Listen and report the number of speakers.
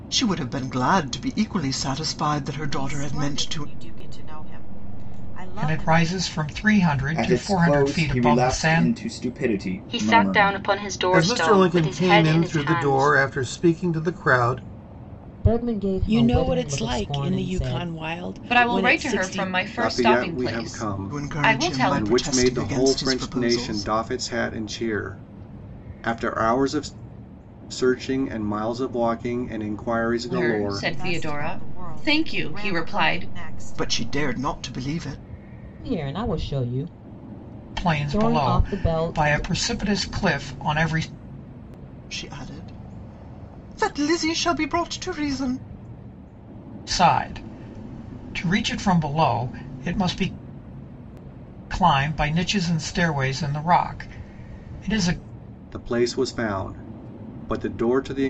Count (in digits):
10